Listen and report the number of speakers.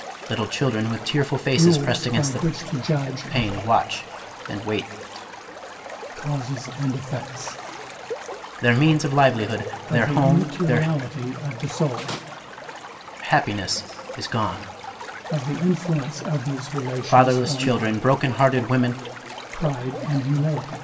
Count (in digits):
2